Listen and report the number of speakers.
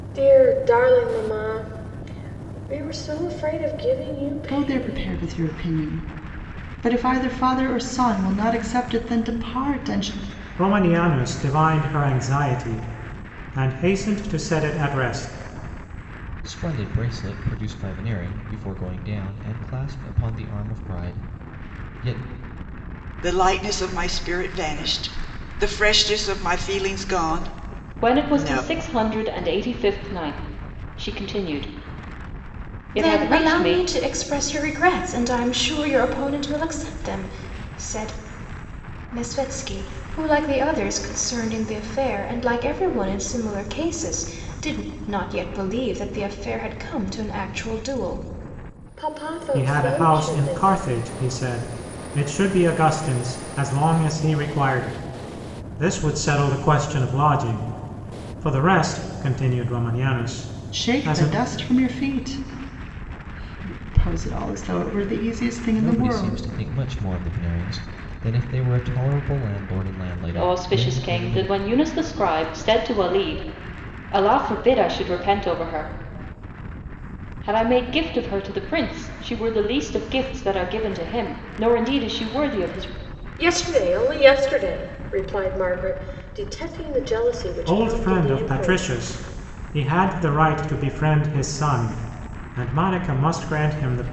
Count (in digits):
7